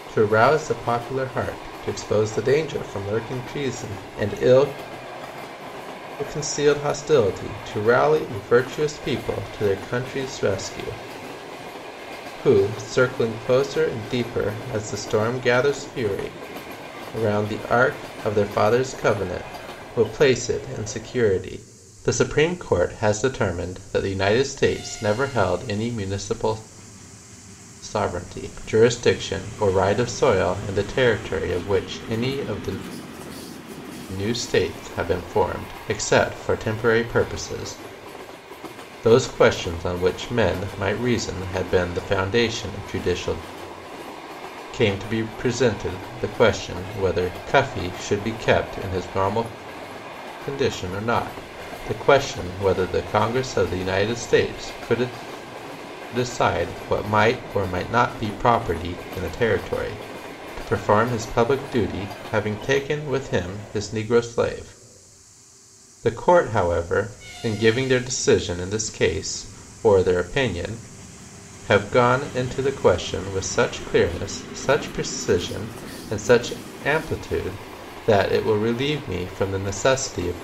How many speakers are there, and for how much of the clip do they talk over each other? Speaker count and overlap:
1, no overlap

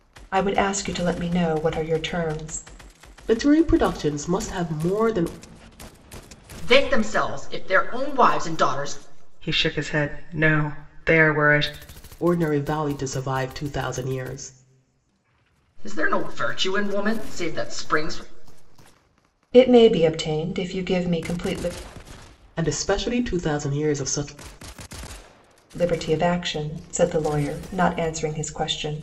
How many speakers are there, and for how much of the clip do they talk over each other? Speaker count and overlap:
4, no overlap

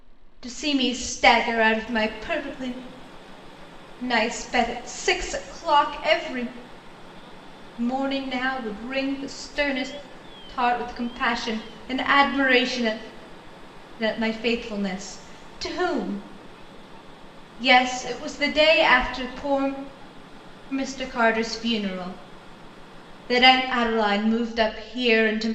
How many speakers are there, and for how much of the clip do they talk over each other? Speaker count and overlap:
1, no overlap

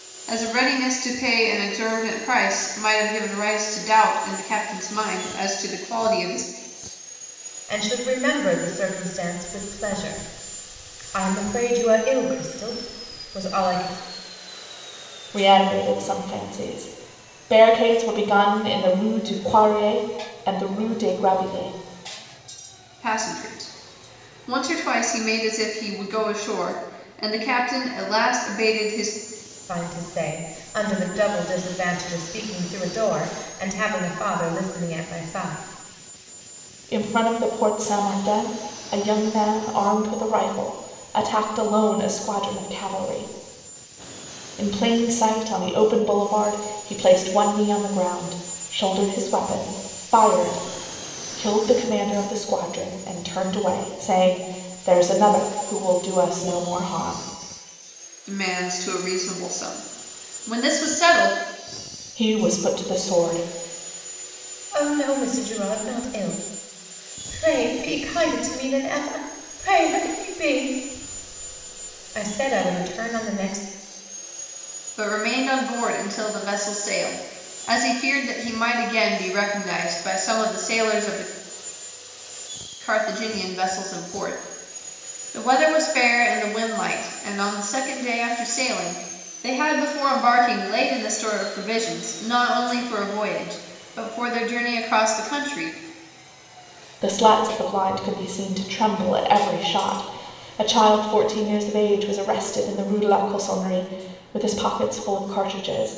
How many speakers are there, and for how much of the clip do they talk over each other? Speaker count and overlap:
3, no overlap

